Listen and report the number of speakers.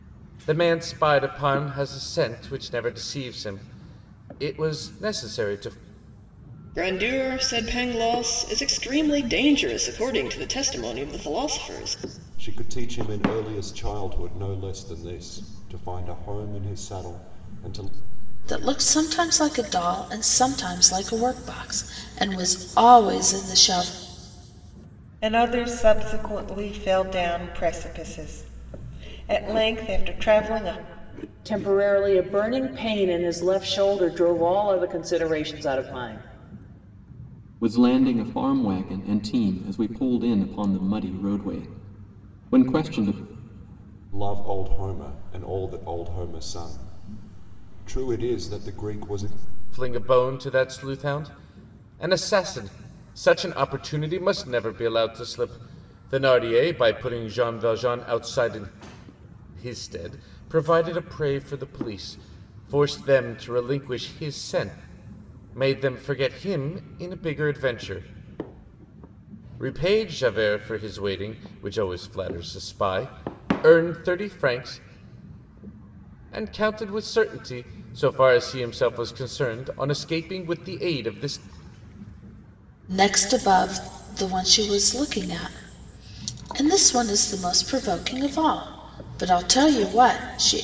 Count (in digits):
7